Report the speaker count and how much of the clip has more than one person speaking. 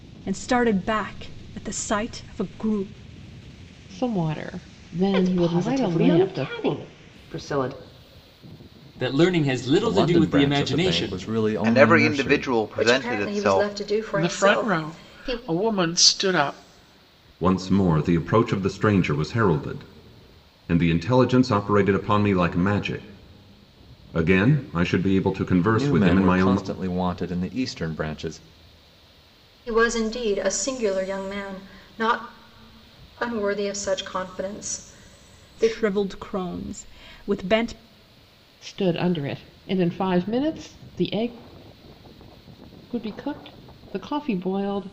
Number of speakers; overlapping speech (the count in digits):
9, about 17%